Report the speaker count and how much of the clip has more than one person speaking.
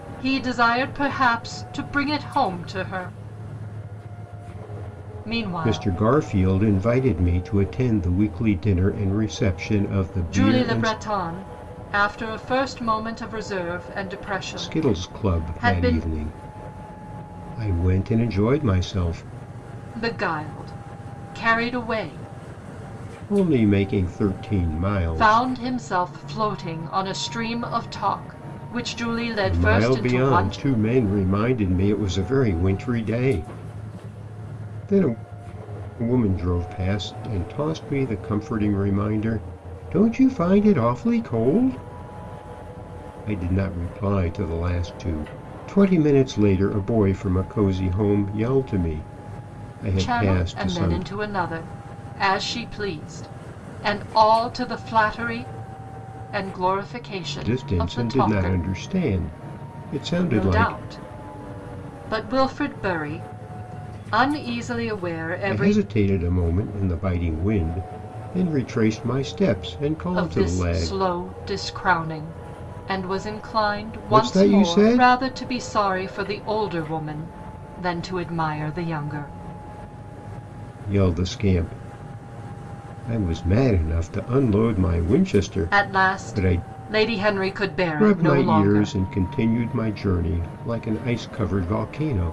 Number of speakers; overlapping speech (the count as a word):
two, about 12%